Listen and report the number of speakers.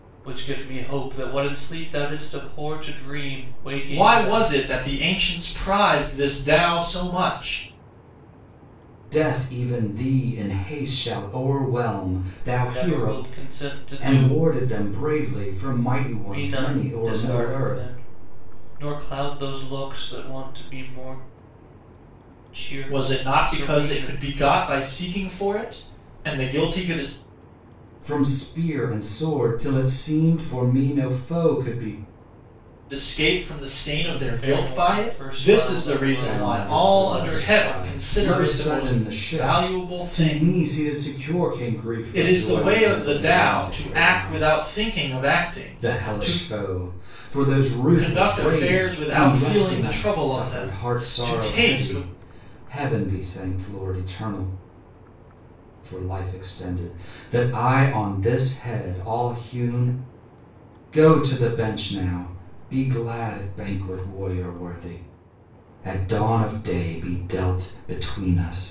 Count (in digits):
3